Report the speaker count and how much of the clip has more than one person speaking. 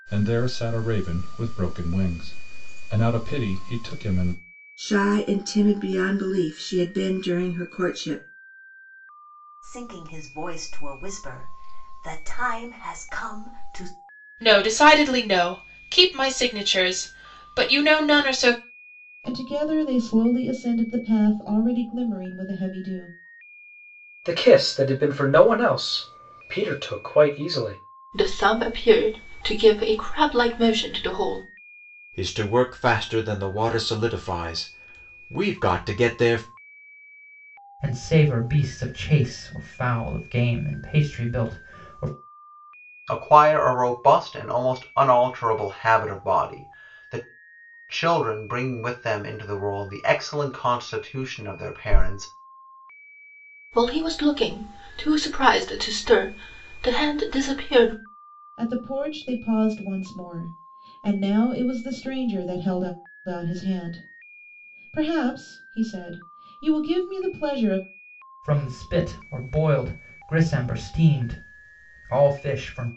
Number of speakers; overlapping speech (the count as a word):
ten, no overlap